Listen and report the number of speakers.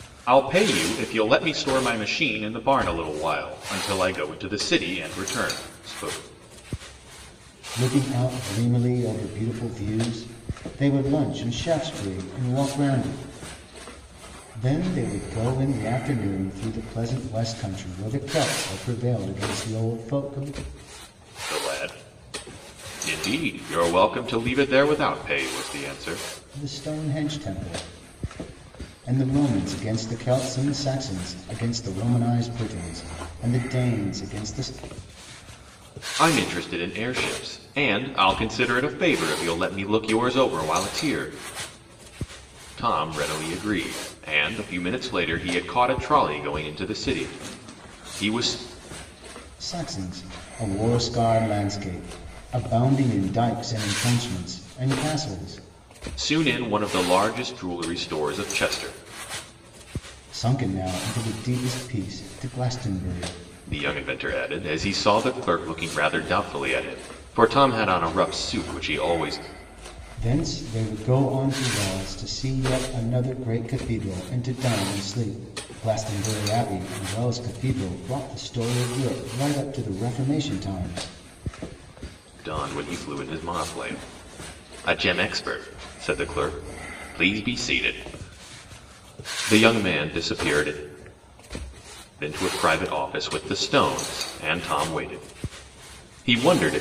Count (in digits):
2